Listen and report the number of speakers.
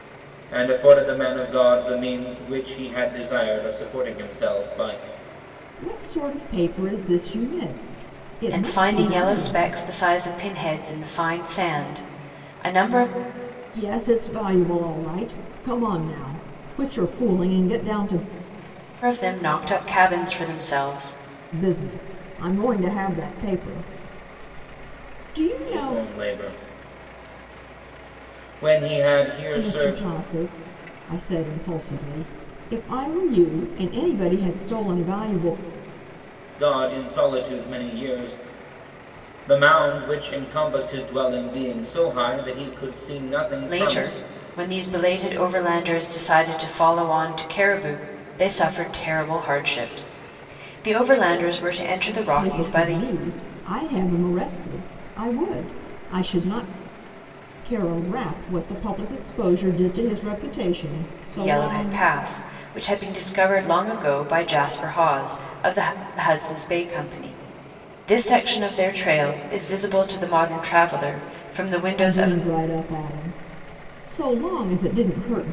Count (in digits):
3